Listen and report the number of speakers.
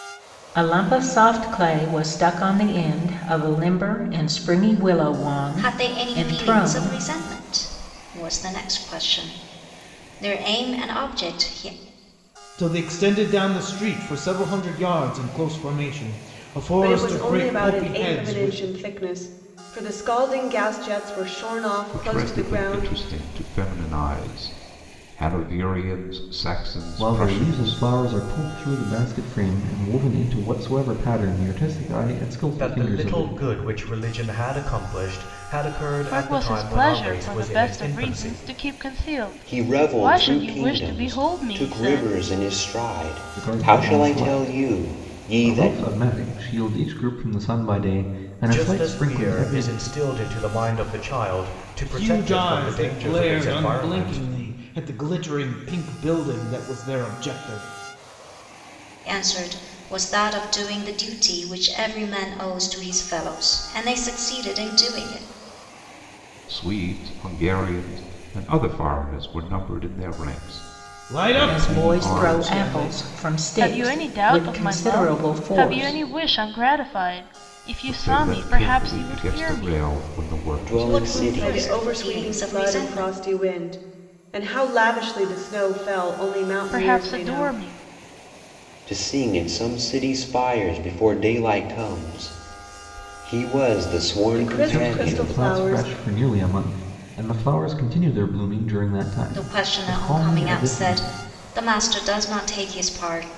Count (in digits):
9